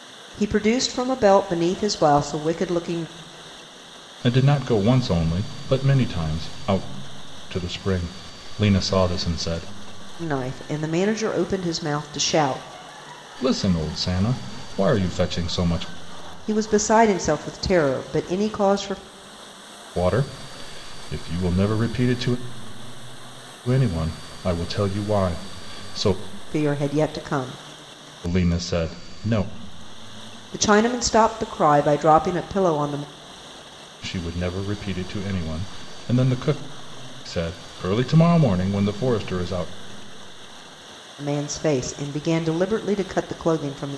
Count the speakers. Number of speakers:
two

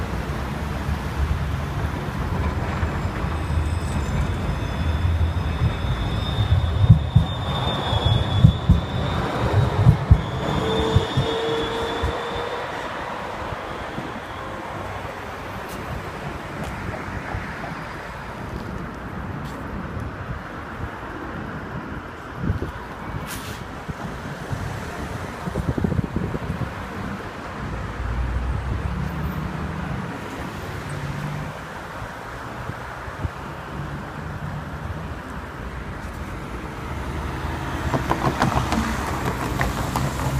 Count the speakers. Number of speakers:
zero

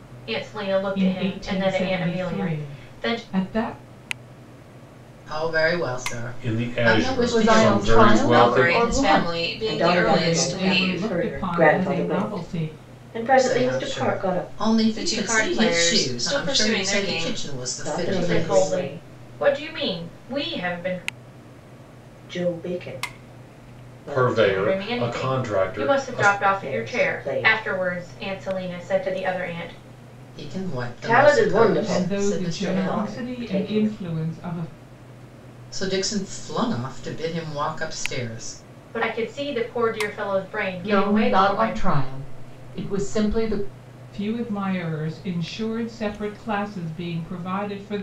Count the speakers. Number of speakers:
seven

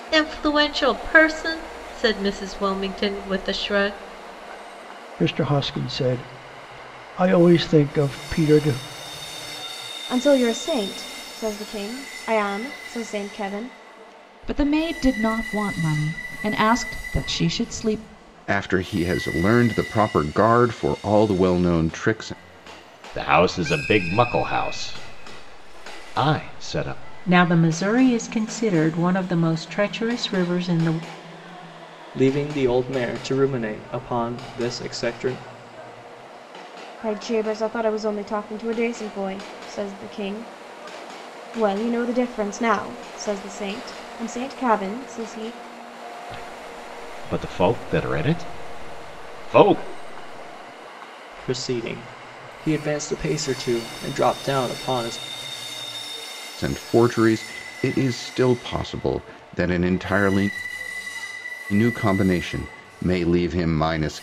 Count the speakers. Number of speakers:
eight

